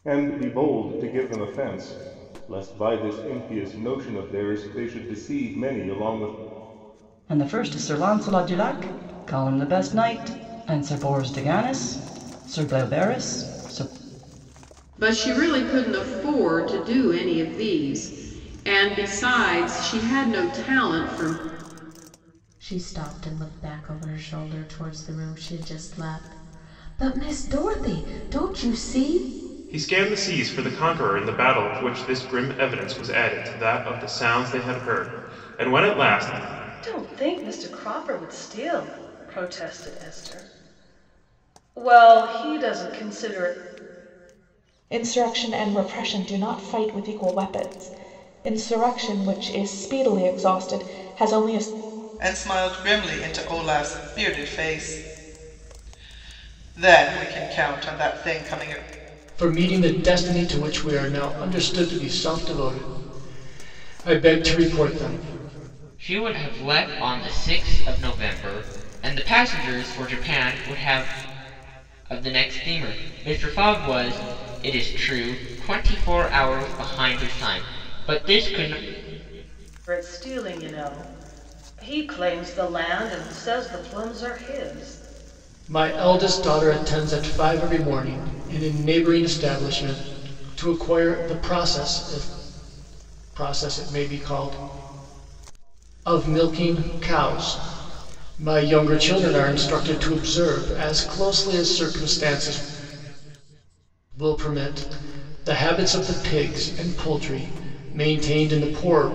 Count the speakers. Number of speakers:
ten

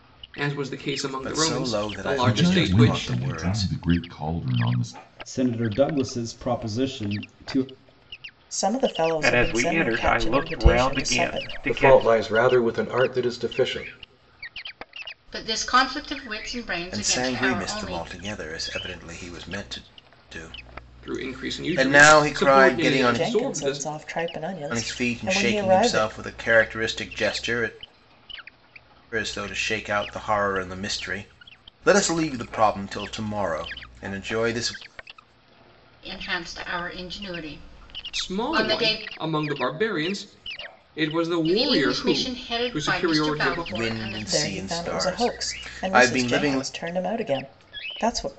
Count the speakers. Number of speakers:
eight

